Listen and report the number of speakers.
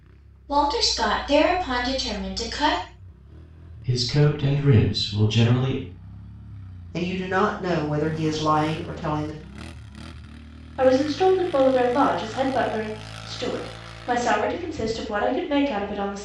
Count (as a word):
four